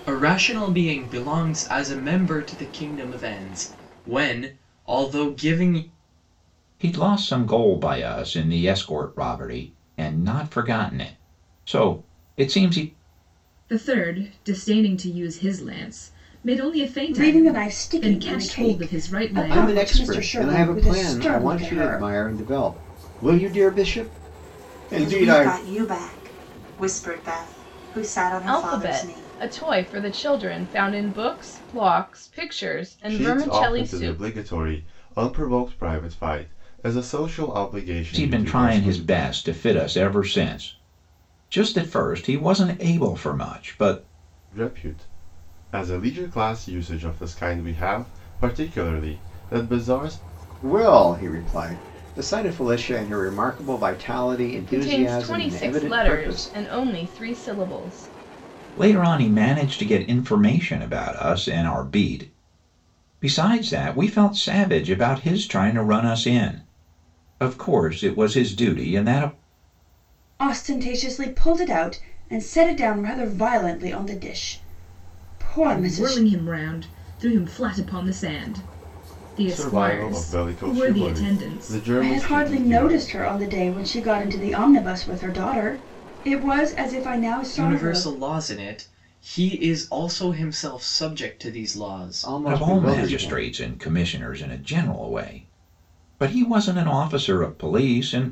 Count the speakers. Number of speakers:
eight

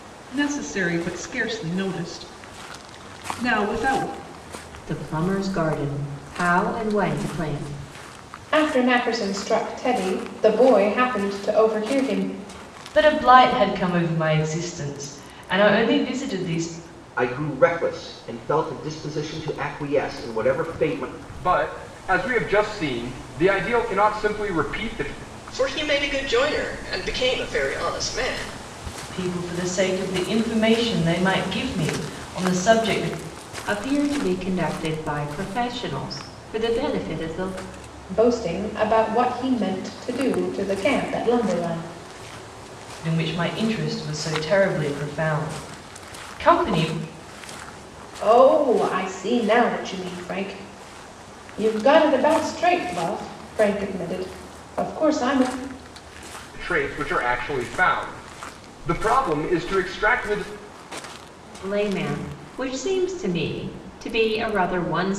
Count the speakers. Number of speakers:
seven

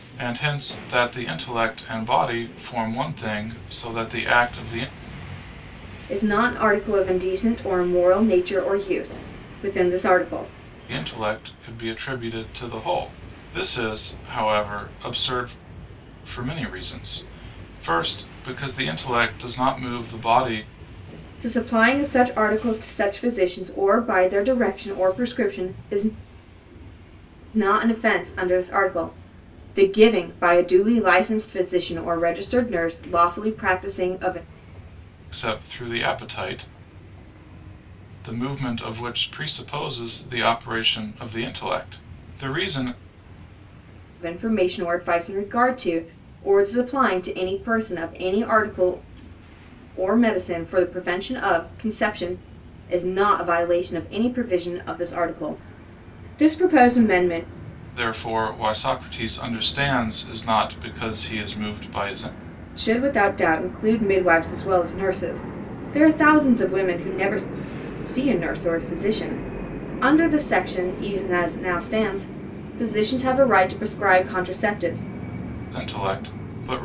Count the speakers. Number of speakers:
two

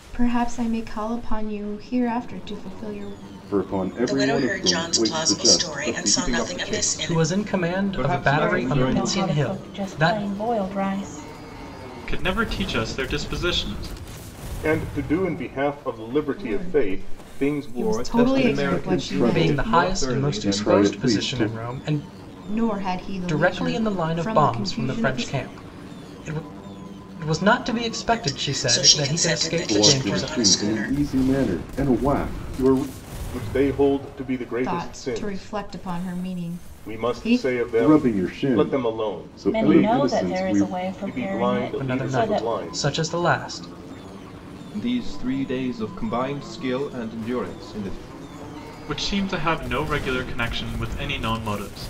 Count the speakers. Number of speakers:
eight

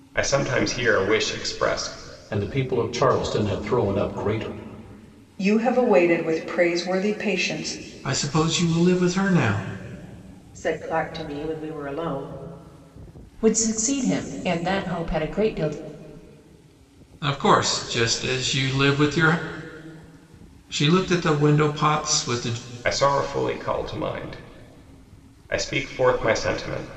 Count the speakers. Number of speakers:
six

